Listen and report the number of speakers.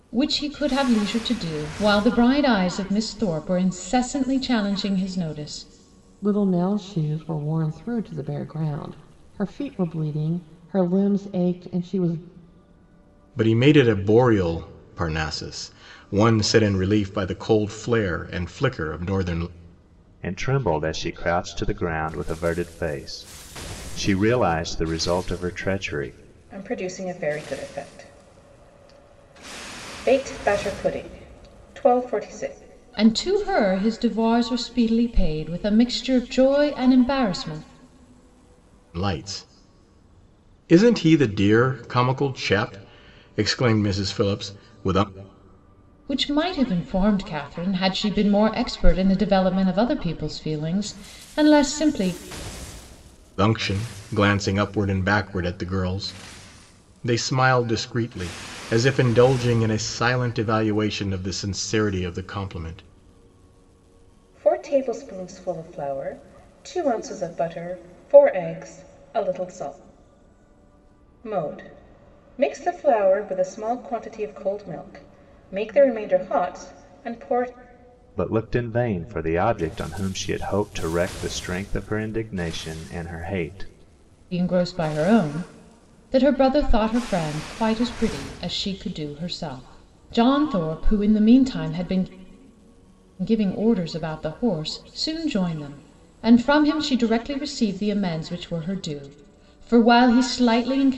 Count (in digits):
5